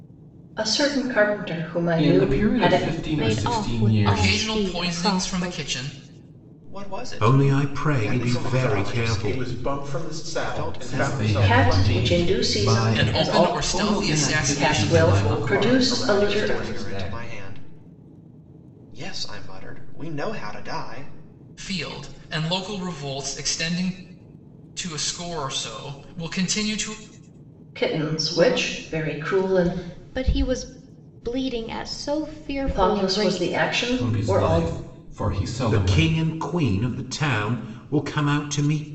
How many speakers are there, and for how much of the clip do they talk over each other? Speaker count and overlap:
seven, about 44%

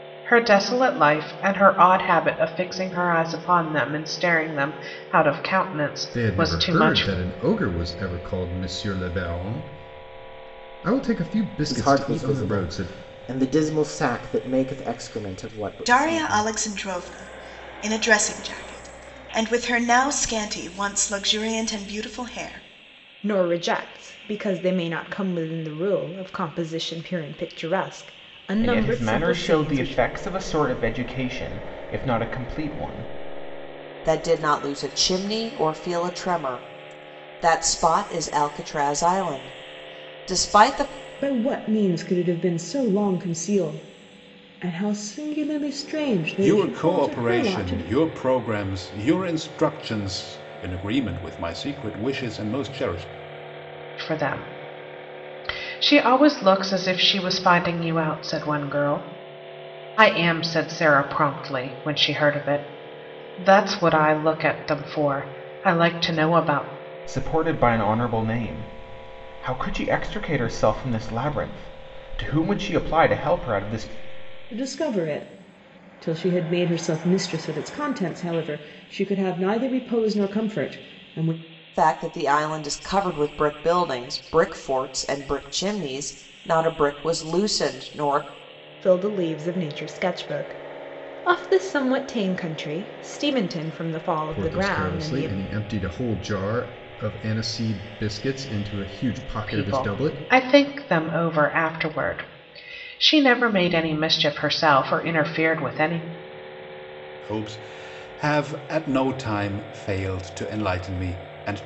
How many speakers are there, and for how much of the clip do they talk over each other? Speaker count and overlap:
nine, about 7%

